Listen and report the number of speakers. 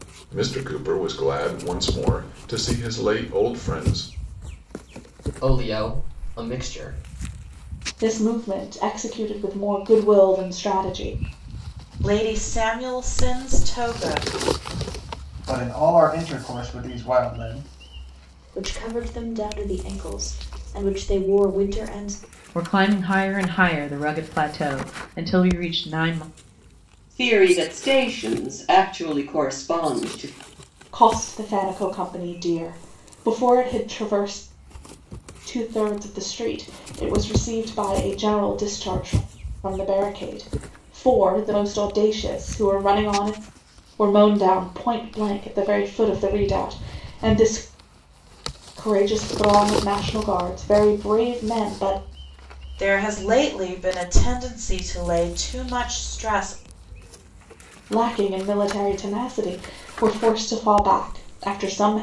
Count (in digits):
8